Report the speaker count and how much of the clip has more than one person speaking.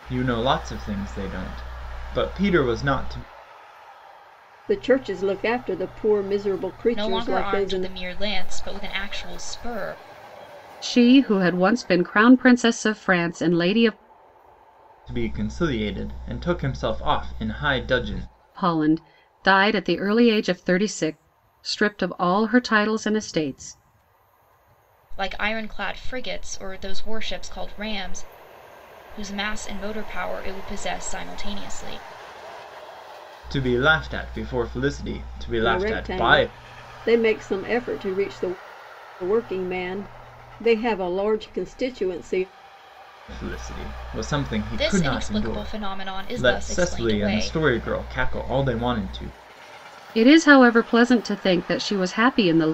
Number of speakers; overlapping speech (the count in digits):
4, about 8%